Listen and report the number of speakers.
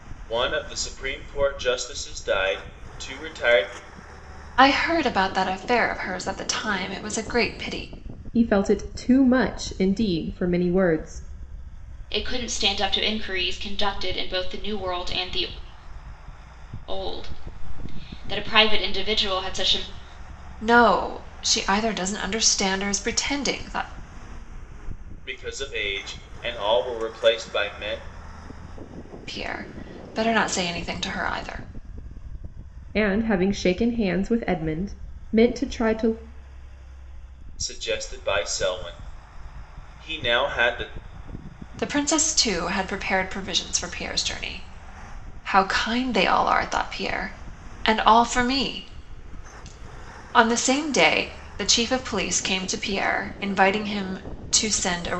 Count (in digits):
4